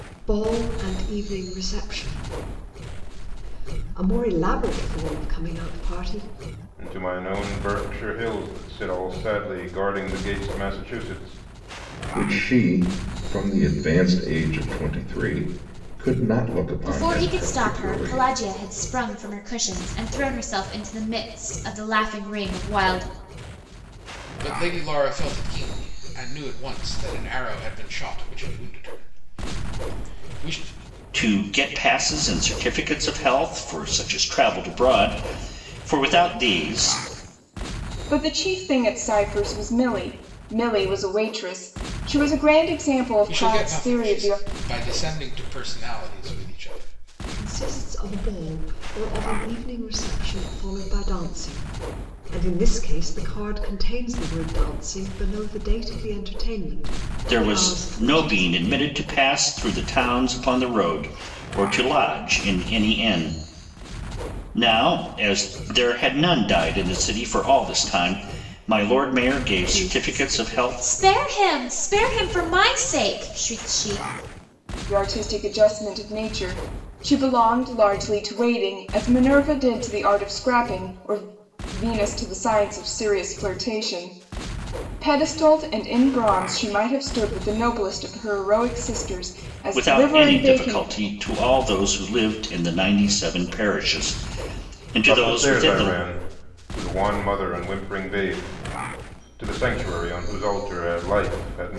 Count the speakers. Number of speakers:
7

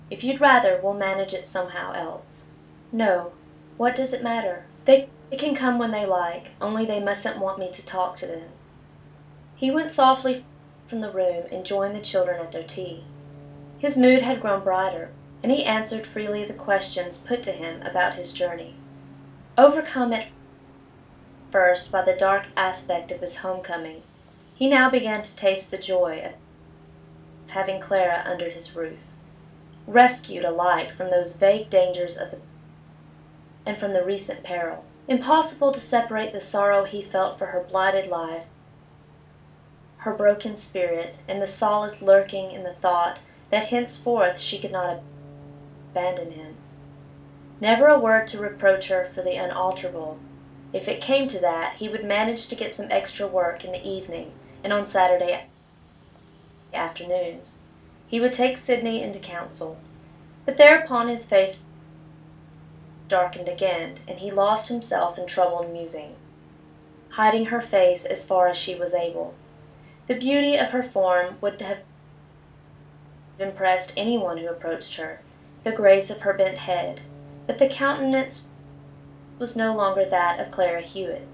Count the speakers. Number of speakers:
1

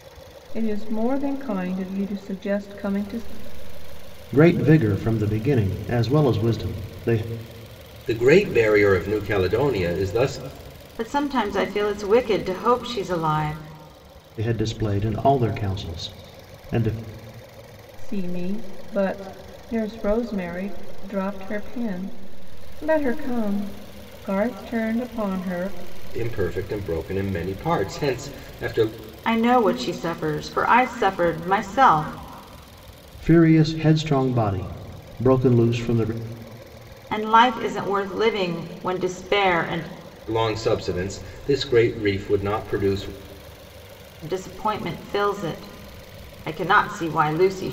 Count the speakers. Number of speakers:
4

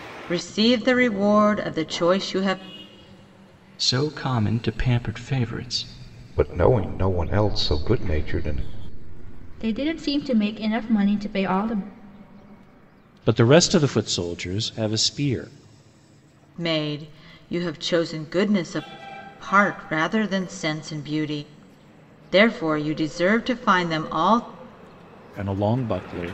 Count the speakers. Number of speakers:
5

